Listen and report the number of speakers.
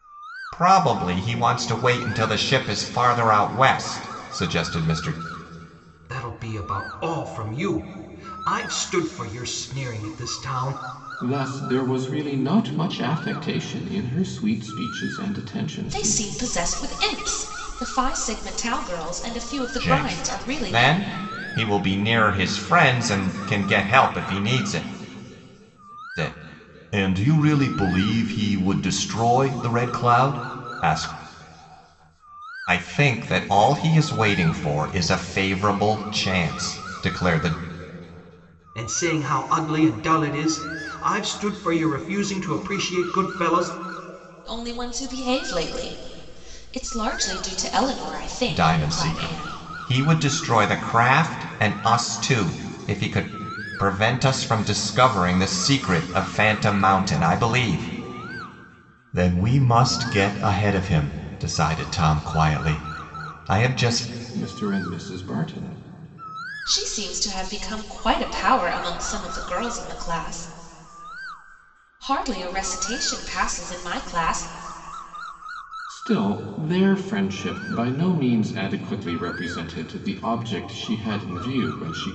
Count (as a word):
four